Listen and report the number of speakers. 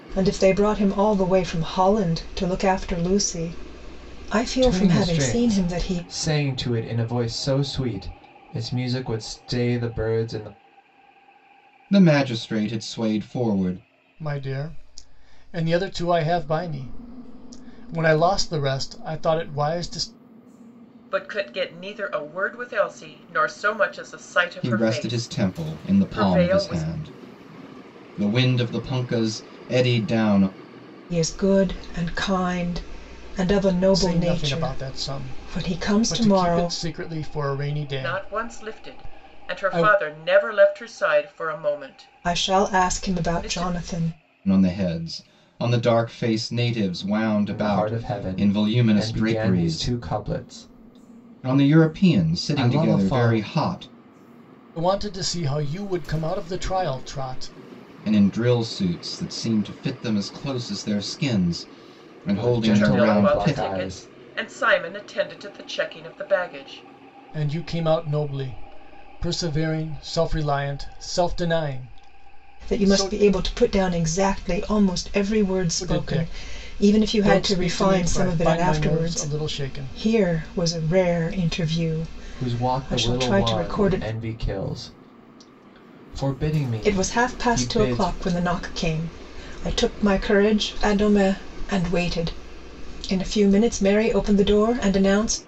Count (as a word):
five